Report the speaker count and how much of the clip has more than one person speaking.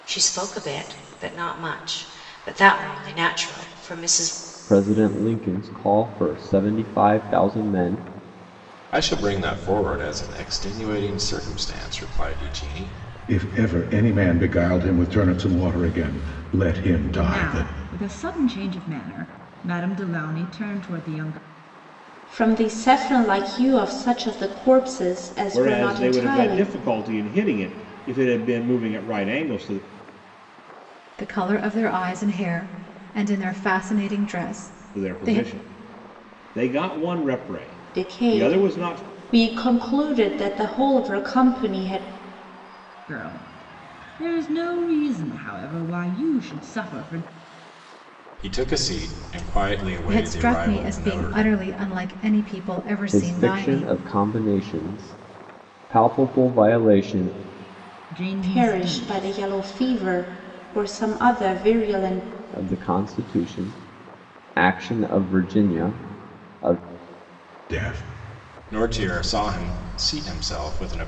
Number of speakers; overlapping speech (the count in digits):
8, about 9%